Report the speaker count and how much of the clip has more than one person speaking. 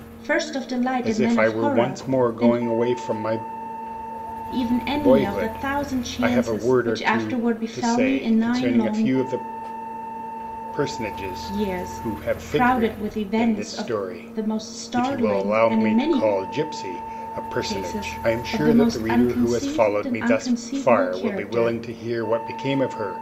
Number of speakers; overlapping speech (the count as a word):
two, about 59%